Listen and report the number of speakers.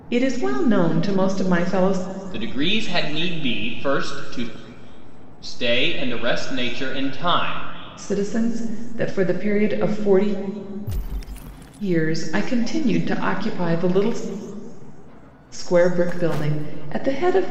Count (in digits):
2